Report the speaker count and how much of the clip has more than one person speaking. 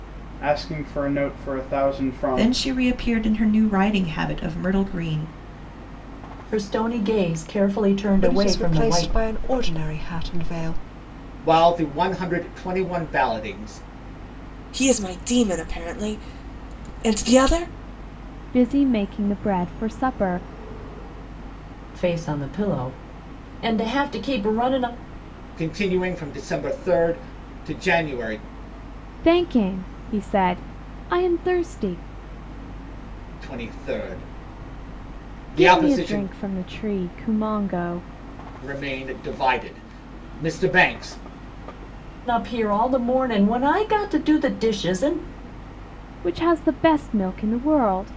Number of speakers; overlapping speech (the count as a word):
seven, about 5%